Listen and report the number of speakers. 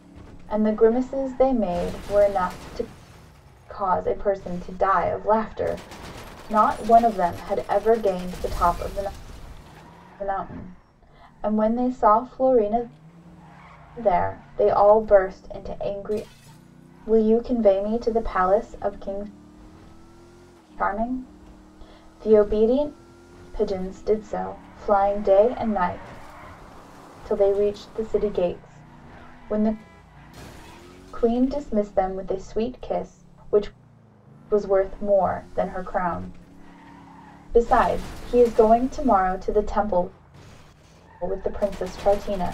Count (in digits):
1